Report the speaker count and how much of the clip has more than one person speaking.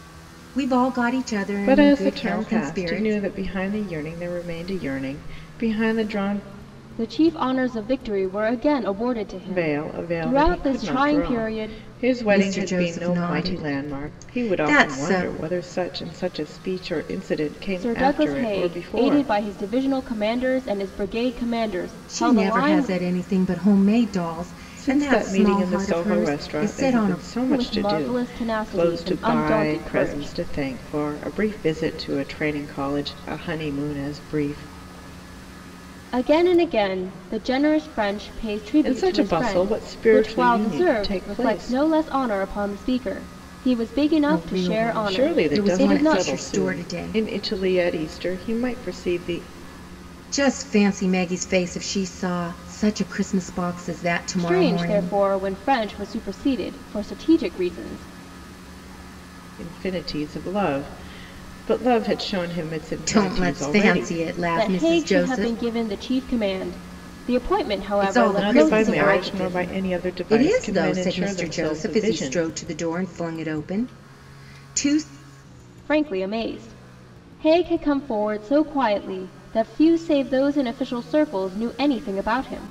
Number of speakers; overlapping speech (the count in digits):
3, about 33%